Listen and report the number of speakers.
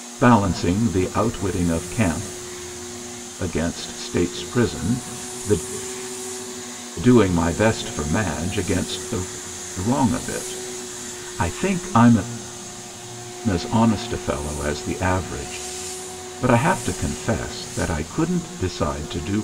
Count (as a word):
one